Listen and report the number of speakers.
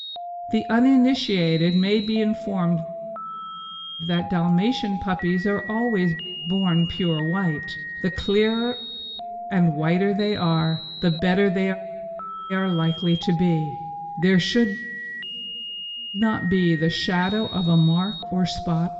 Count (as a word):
one